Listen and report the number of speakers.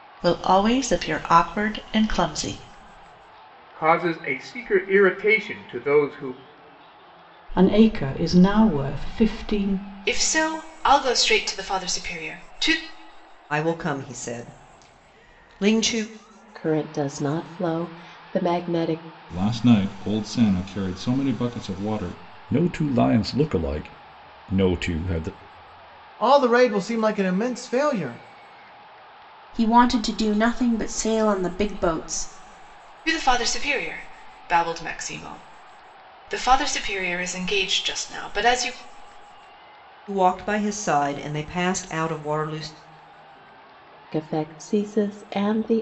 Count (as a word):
ten